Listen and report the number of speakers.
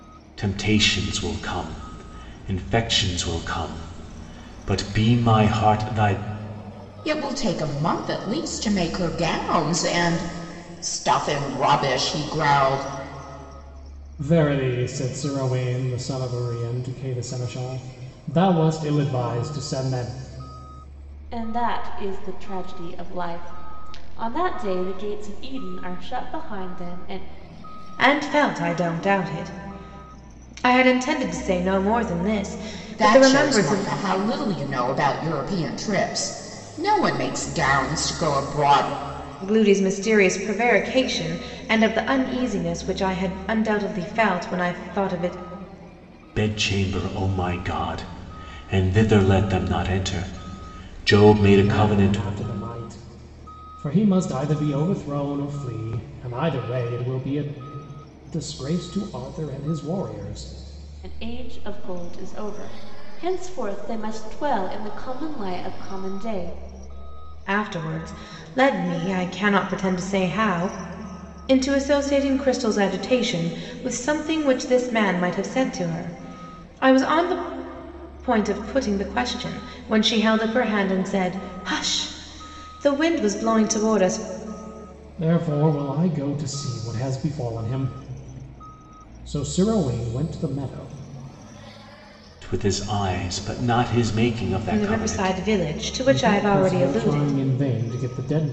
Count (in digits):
5